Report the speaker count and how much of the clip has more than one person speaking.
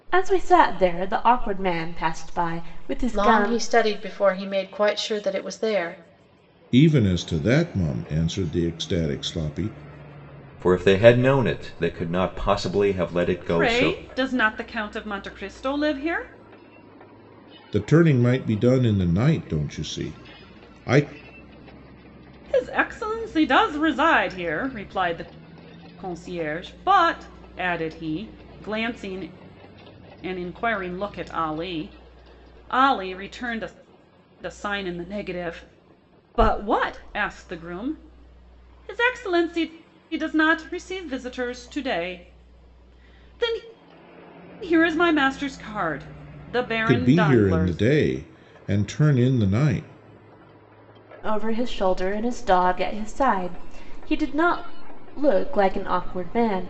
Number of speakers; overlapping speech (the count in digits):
5, about 4%